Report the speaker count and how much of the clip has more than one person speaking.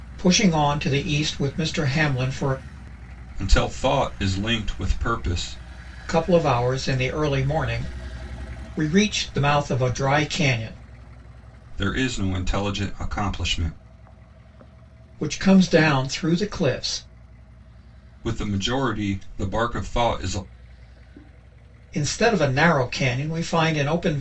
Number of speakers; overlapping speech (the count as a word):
two, no overlap